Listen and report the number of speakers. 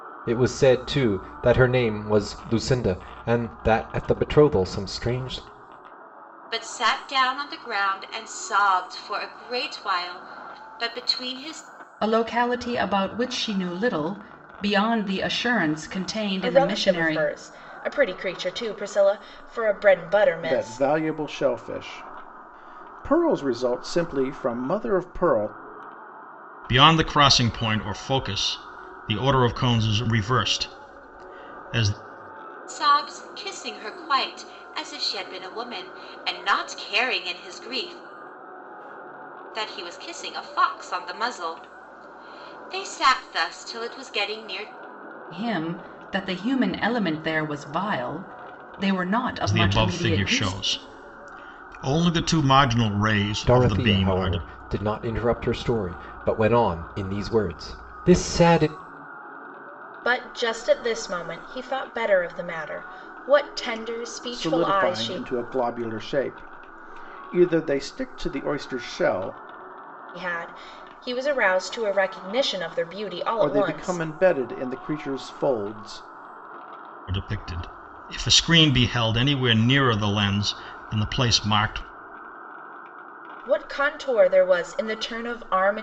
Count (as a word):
six